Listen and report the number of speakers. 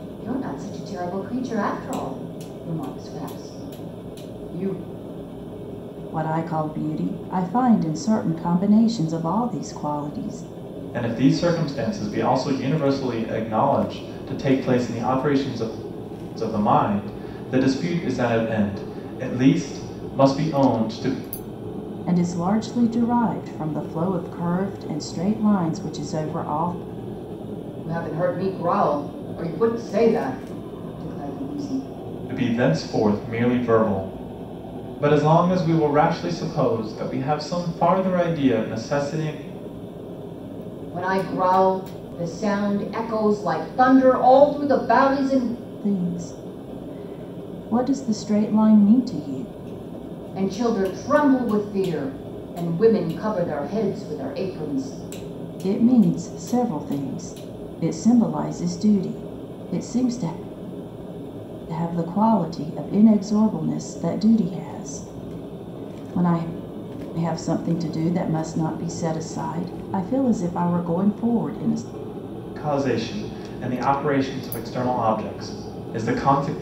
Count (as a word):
three